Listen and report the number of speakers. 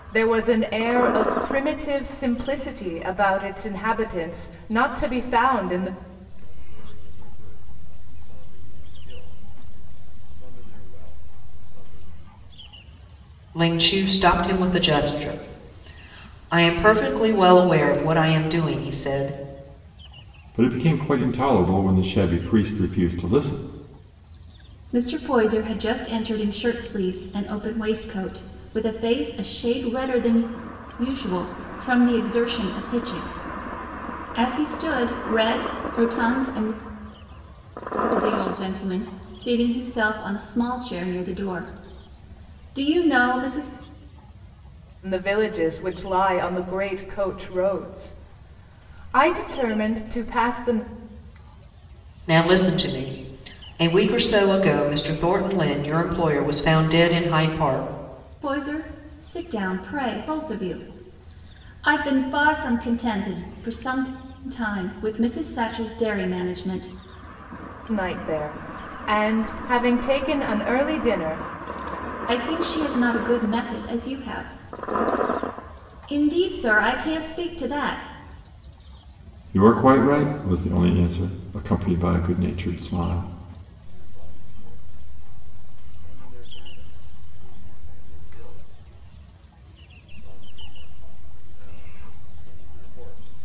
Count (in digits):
5